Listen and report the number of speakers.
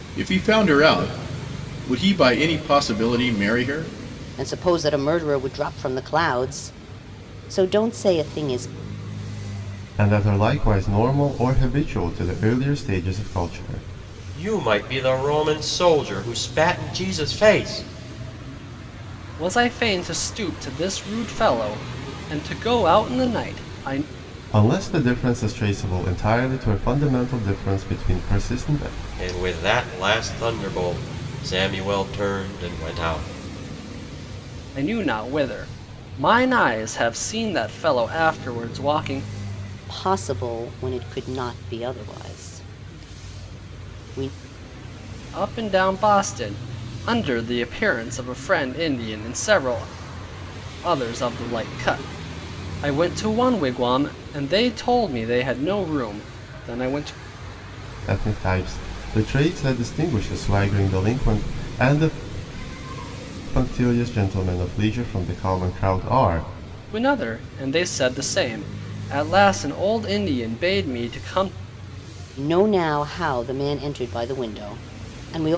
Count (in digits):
5